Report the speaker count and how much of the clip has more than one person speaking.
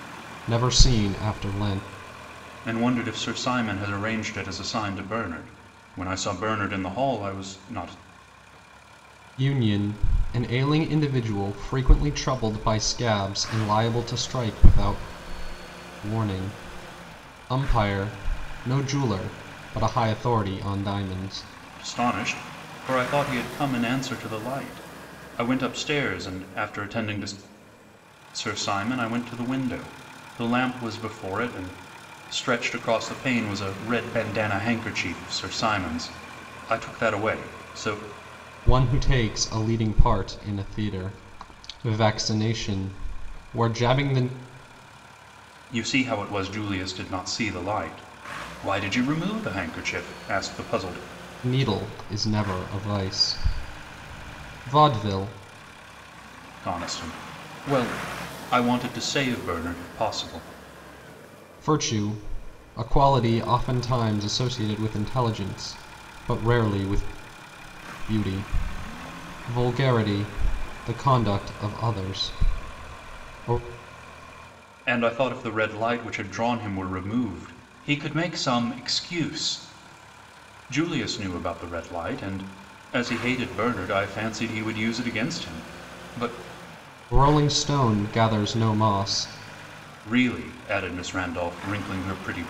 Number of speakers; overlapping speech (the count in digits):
2, no overlap